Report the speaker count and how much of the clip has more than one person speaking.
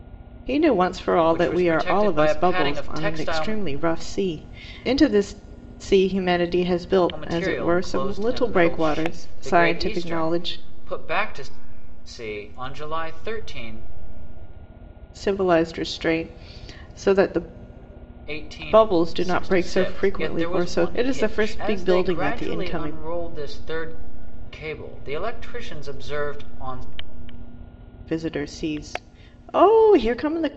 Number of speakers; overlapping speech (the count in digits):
2, about 33%